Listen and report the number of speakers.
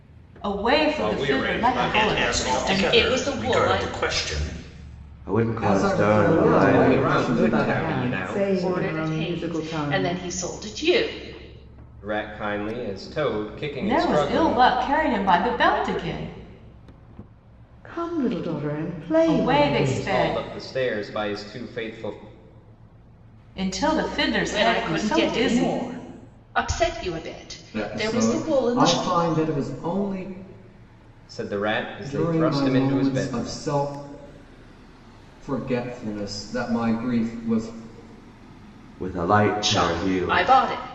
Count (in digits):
7